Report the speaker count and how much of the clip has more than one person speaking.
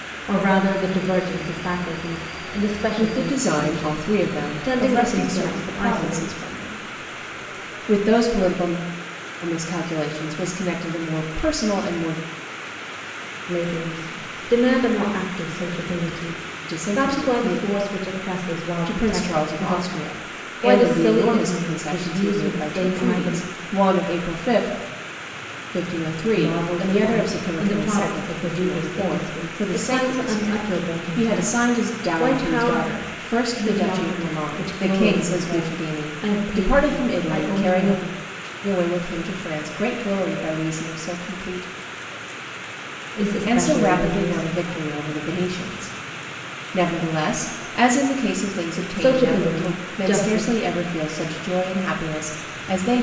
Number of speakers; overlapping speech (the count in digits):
2, about 41%